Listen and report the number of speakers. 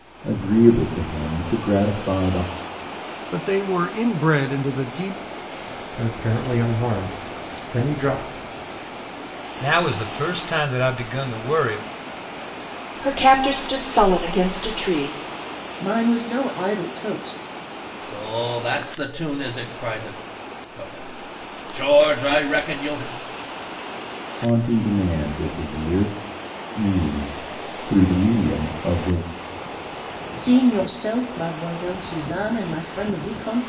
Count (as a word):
seven